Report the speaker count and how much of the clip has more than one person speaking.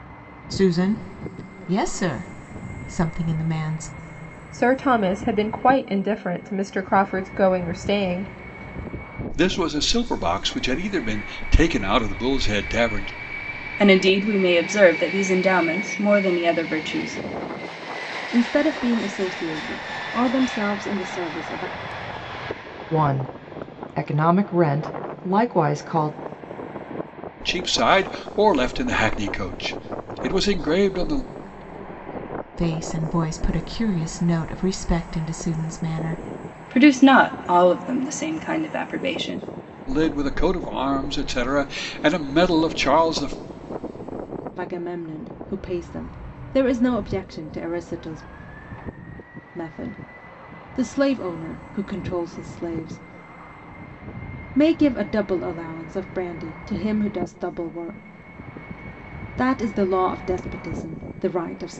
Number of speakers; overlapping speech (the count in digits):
6, no overlap